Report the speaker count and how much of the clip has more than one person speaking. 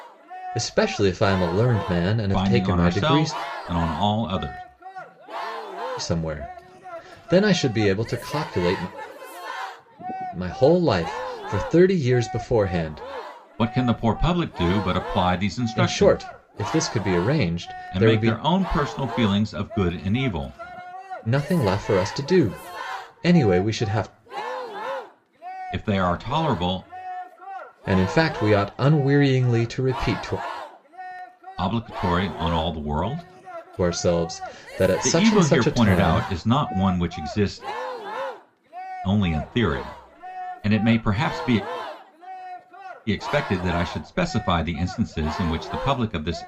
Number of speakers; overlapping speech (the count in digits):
2, about 8%